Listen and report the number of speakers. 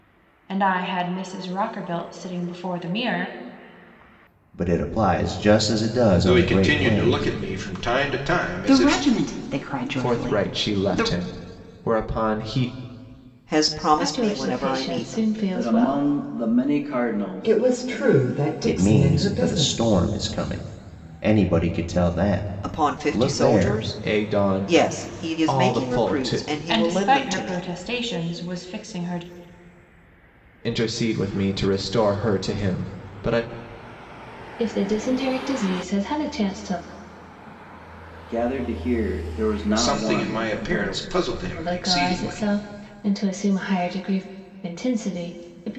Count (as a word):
nine